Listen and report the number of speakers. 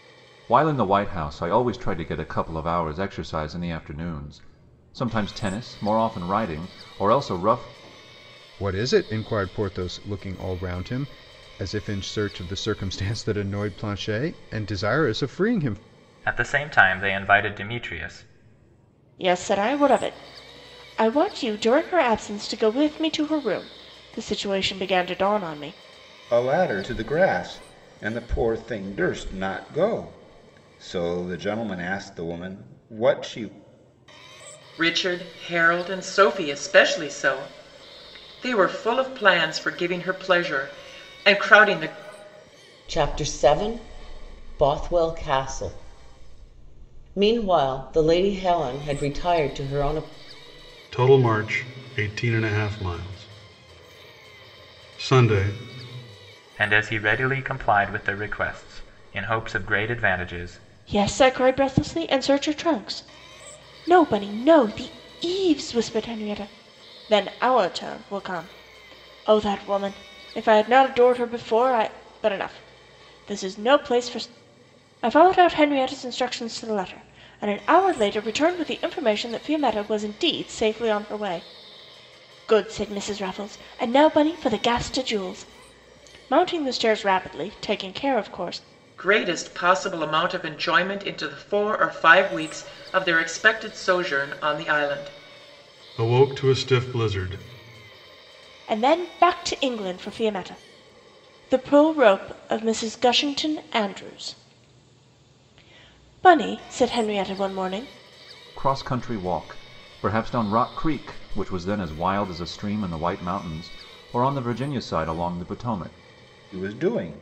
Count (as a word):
eight